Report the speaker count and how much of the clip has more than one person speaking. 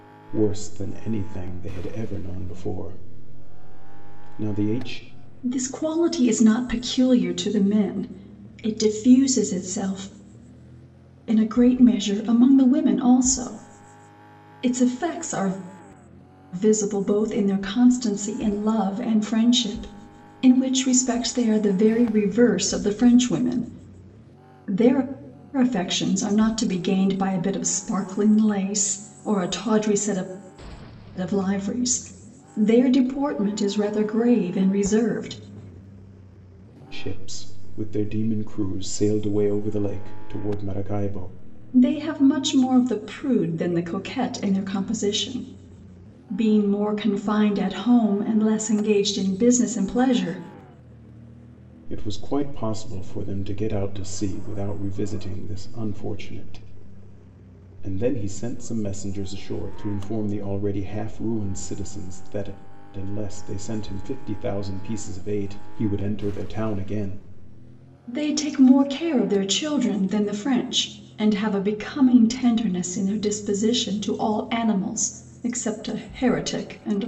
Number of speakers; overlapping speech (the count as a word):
two, no overlap